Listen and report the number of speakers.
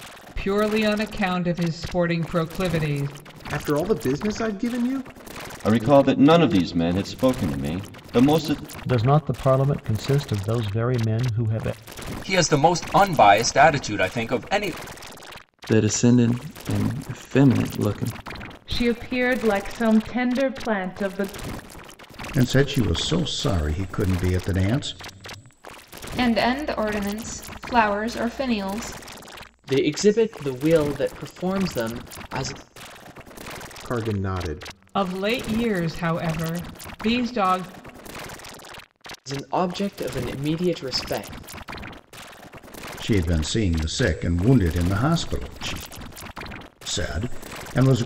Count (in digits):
10